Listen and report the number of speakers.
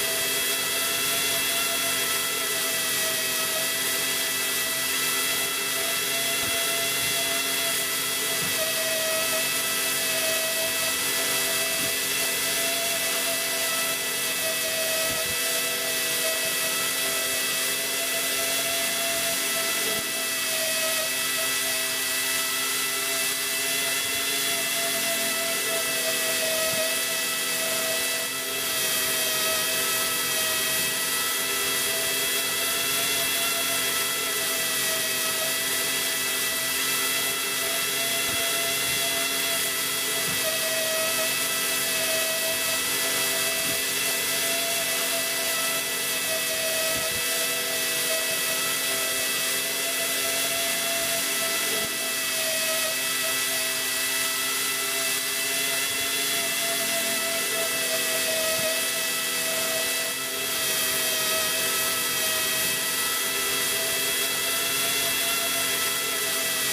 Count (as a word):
zero